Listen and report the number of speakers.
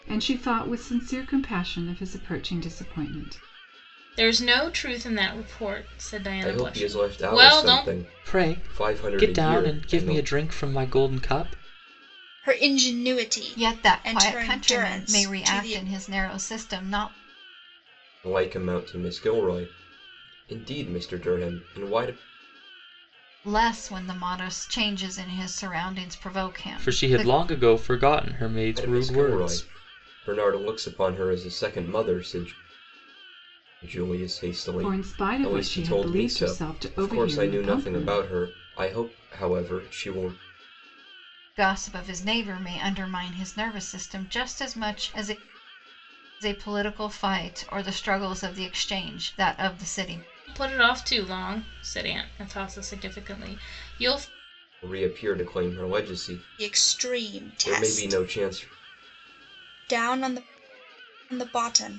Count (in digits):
6